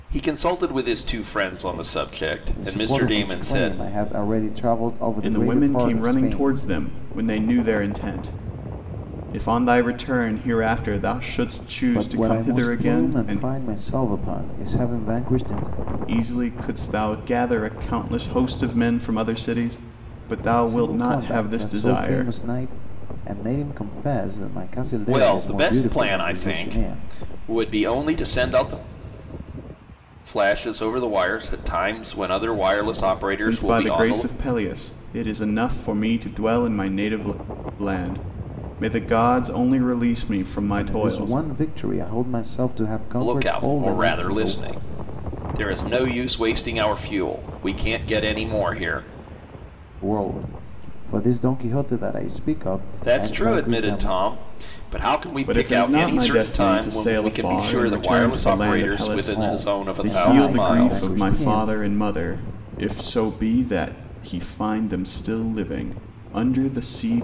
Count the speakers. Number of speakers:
3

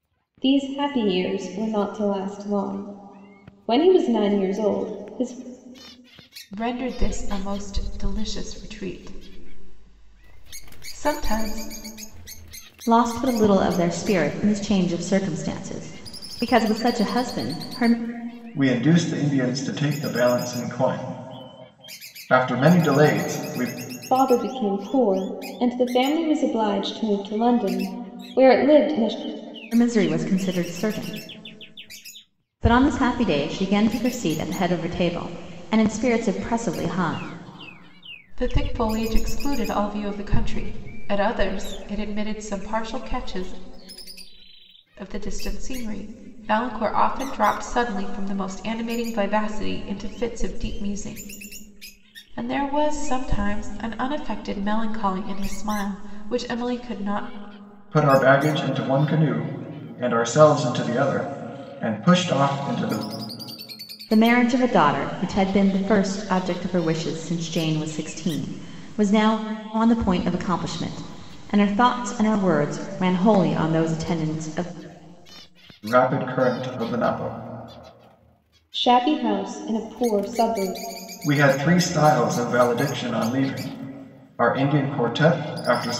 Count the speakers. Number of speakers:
4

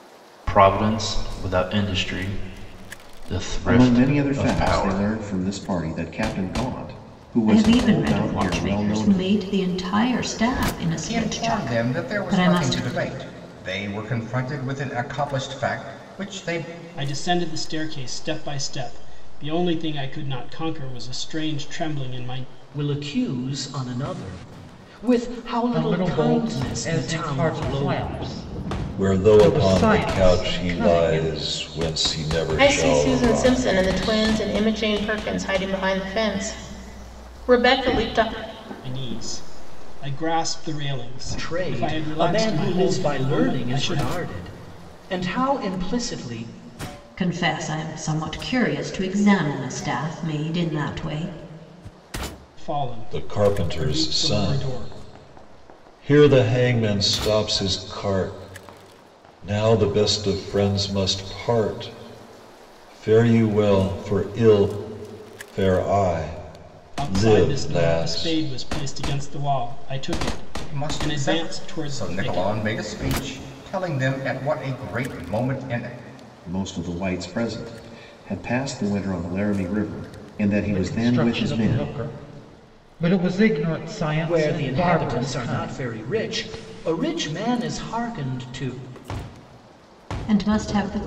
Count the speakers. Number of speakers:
9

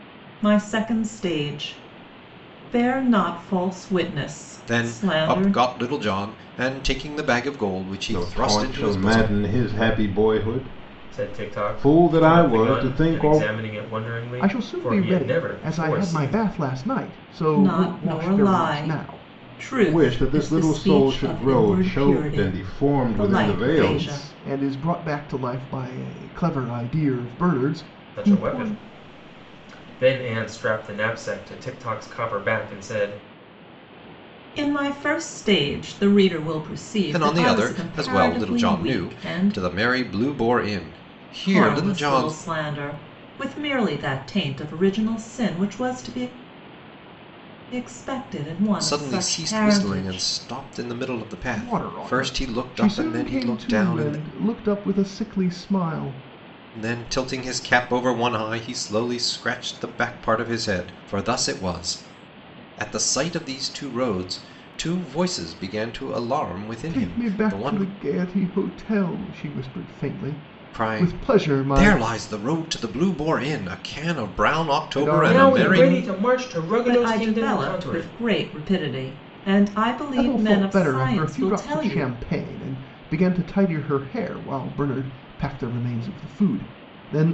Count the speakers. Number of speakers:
5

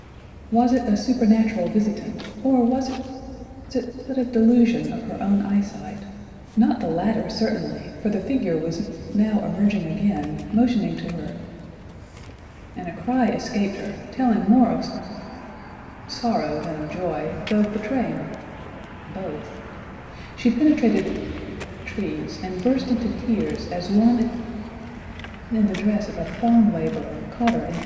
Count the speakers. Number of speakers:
1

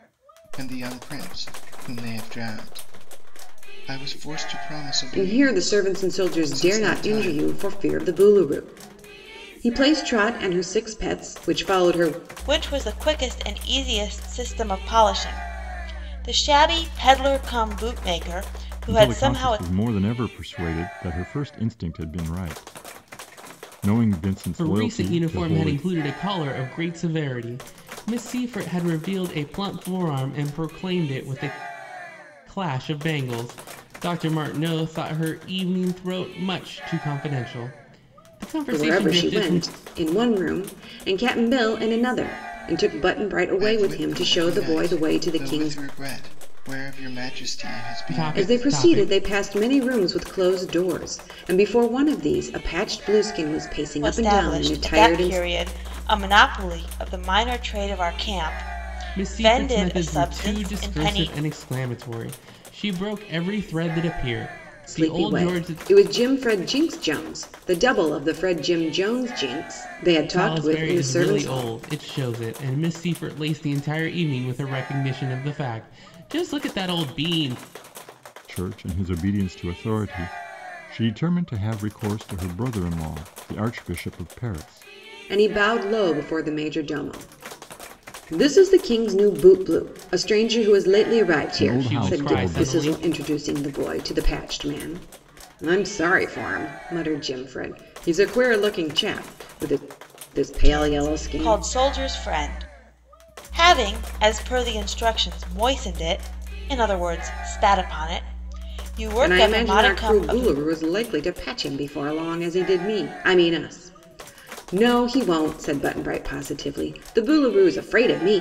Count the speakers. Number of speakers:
5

